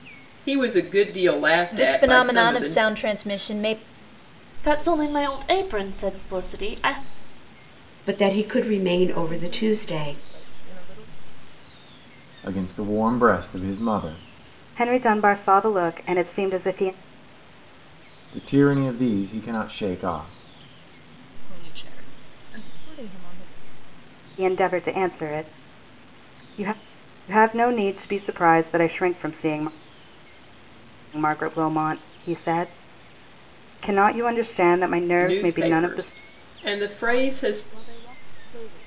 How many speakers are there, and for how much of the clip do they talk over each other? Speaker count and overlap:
seven, about 10%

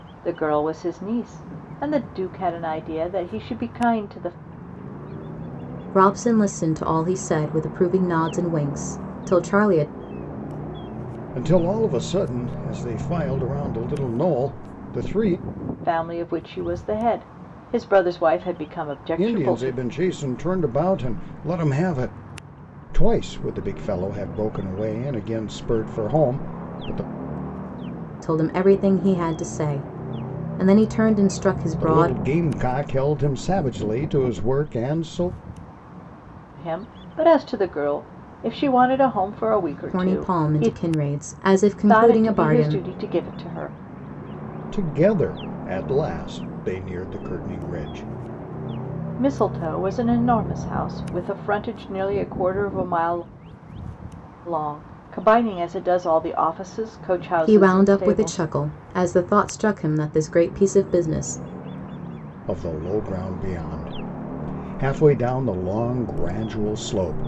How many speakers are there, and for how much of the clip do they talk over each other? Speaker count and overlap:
three, about 6%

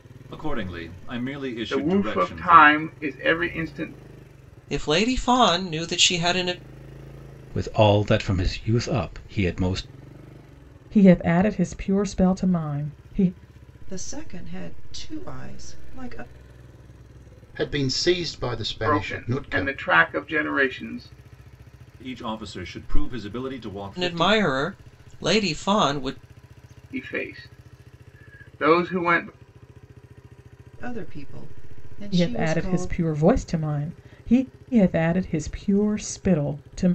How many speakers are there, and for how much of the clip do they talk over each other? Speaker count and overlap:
seven, about 9%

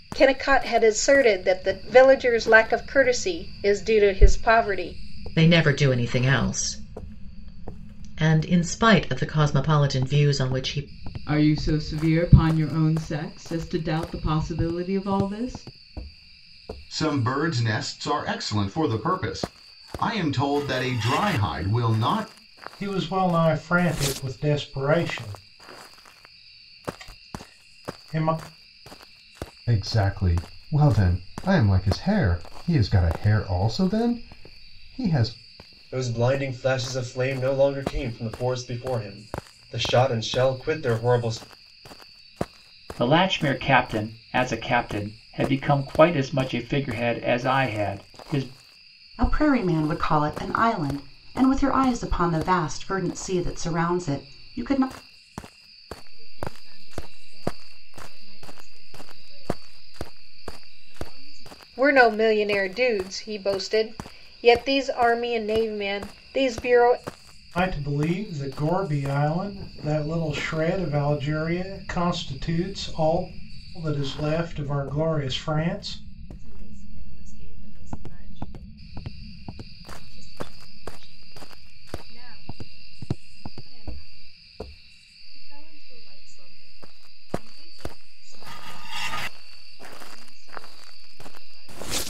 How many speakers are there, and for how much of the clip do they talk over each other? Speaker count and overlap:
ten, no overlap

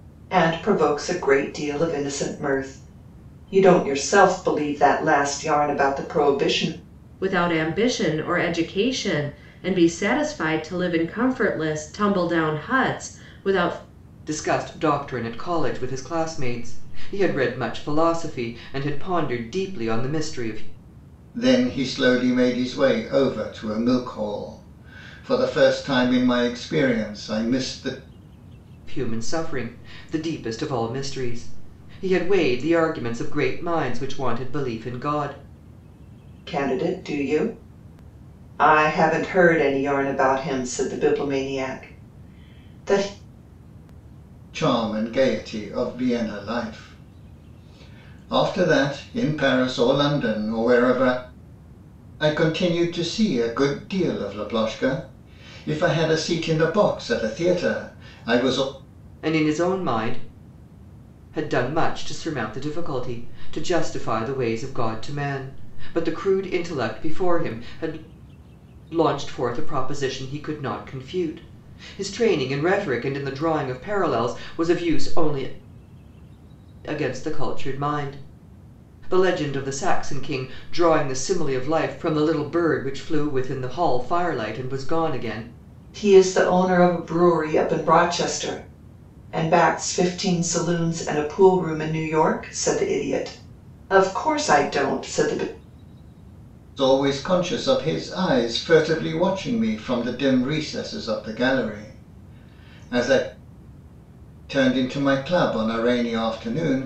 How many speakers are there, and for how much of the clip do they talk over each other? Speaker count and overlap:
four, no overlap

